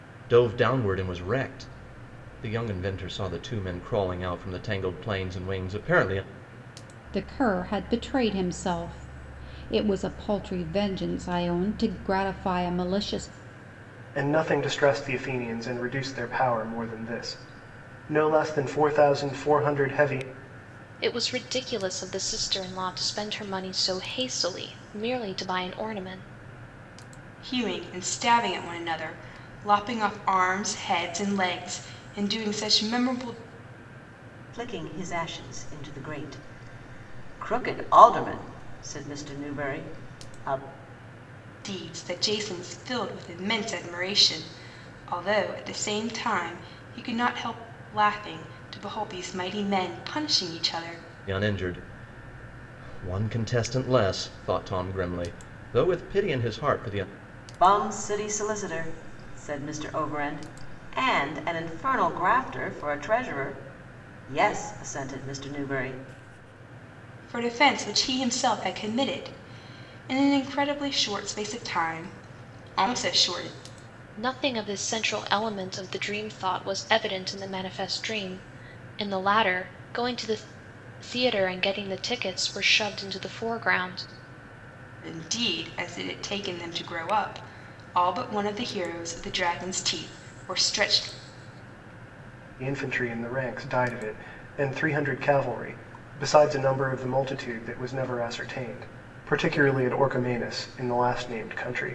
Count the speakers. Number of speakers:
6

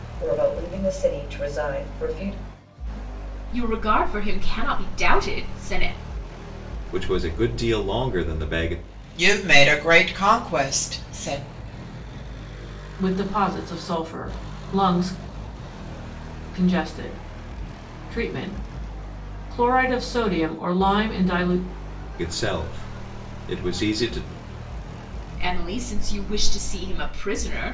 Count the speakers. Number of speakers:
5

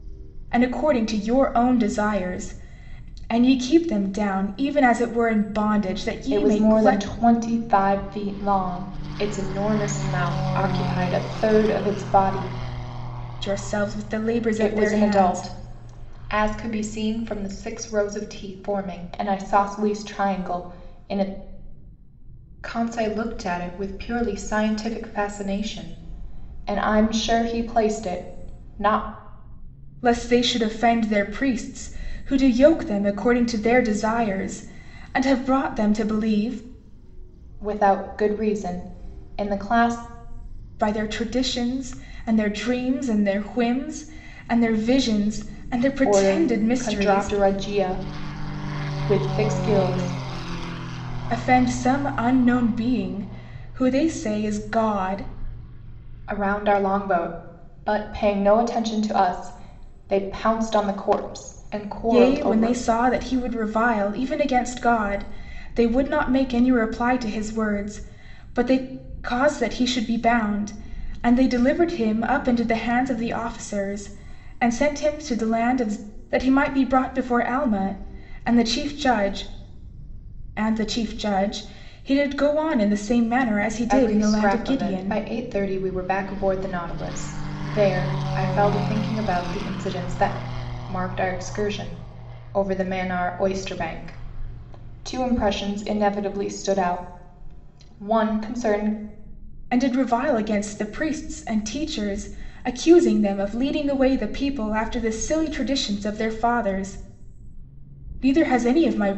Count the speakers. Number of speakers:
2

